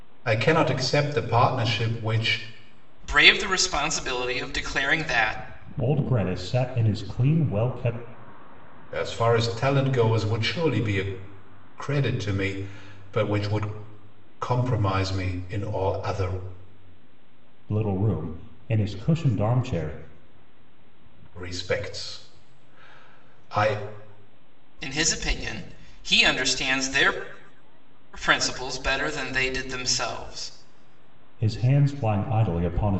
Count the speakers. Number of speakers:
three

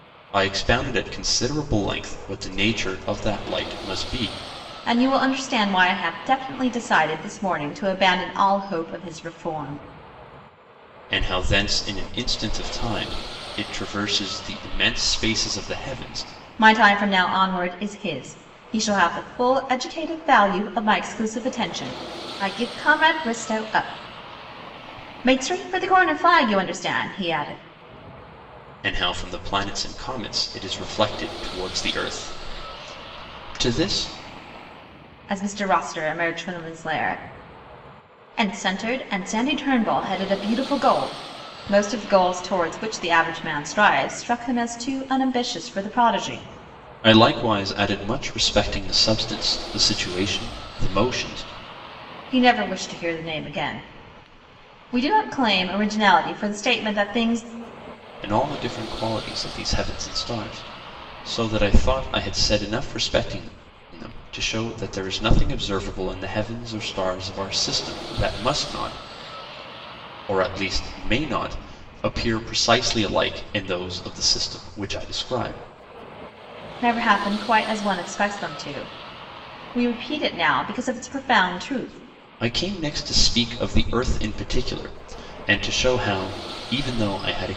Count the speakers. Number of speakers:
two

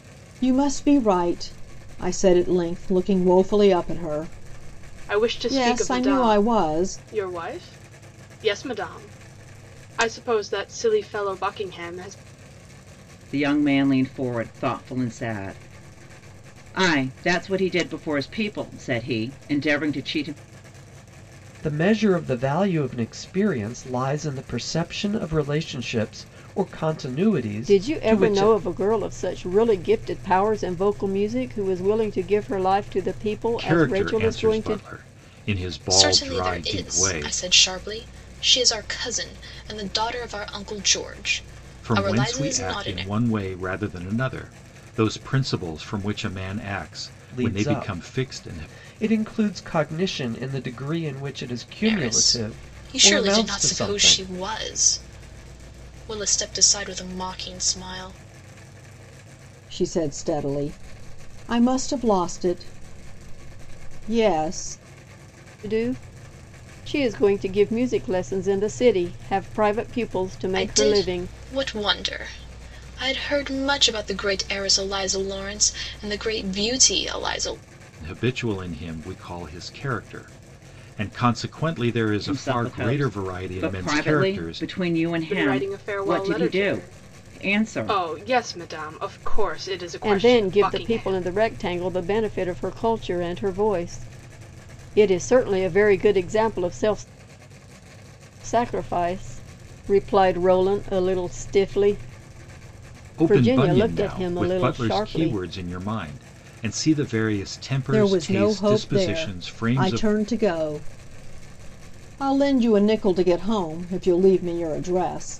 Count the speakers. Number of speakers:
seven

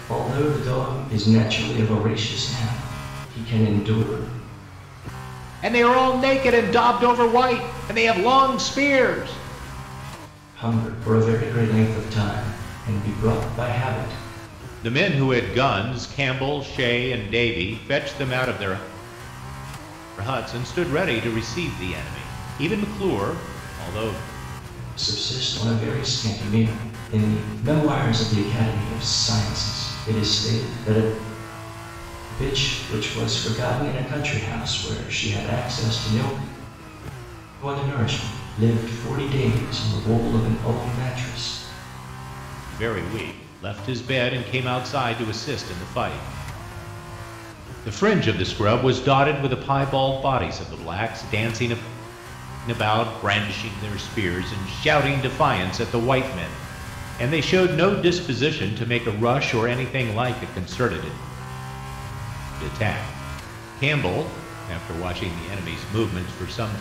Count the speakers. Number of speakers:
two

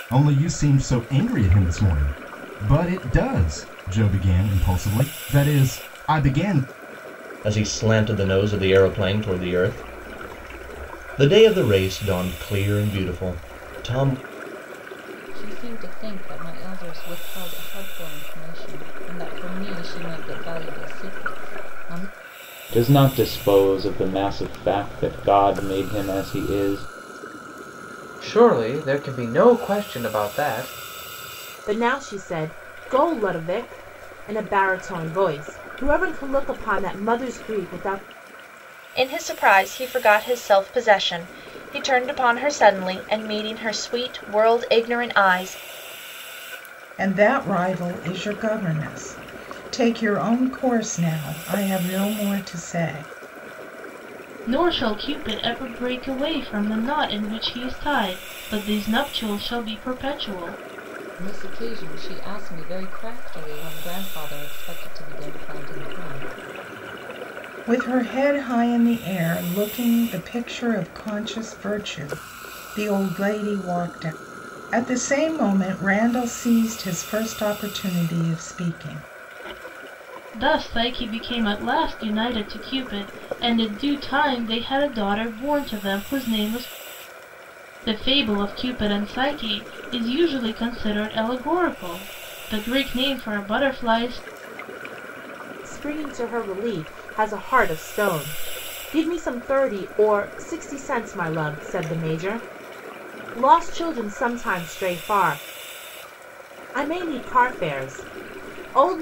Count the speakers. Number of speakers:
nine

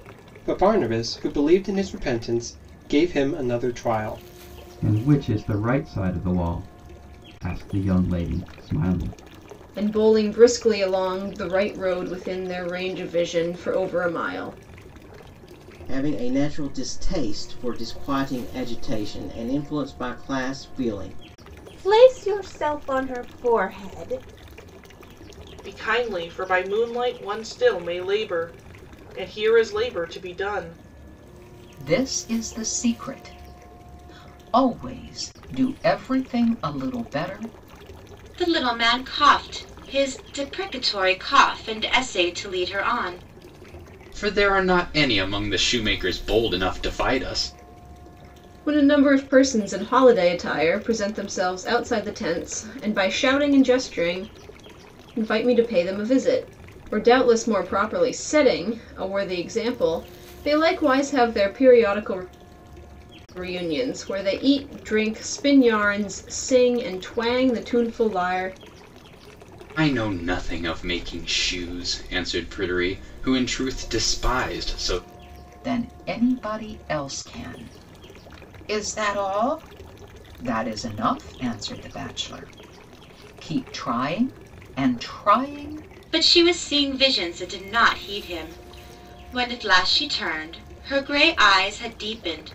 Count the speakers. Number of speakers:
nine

